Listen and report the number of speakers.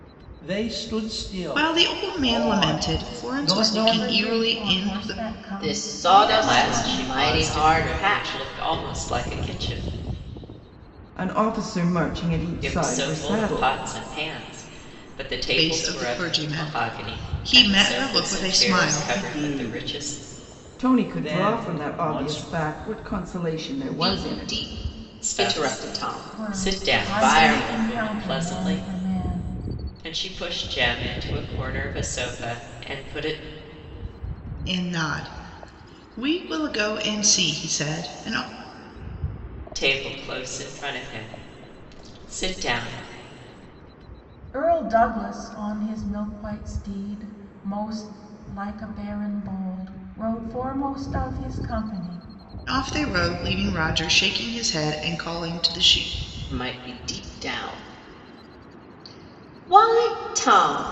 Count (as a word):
six